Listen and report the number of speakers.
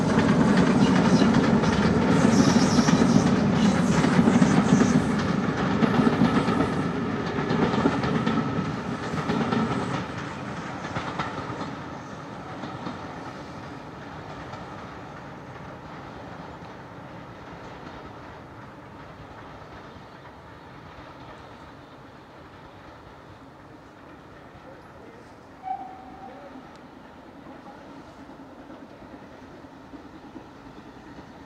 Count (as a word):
zero